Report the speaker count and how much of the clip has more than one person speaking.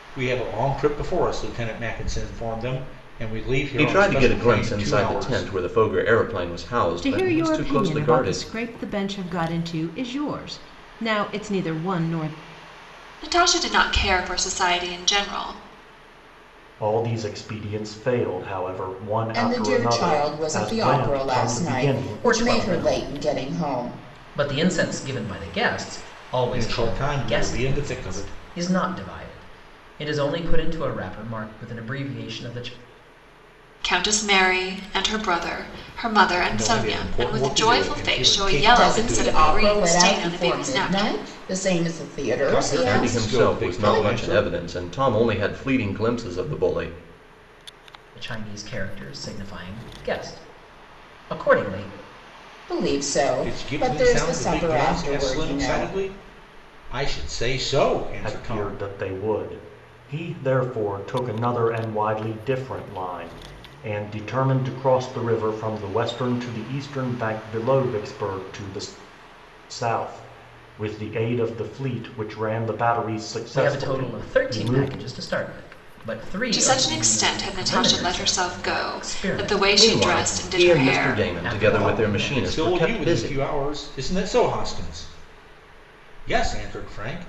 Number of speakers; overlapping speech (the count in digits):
7, about 33%